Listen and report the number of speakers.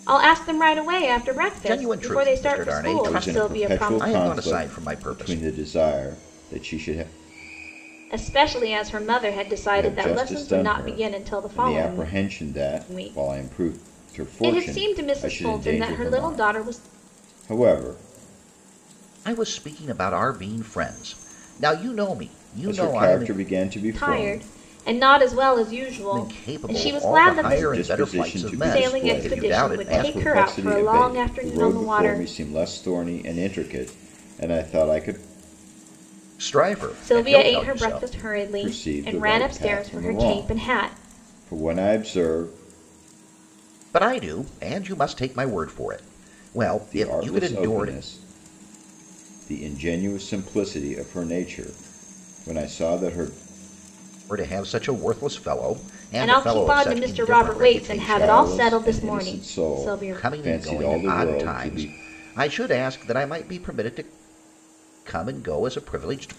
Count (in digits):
3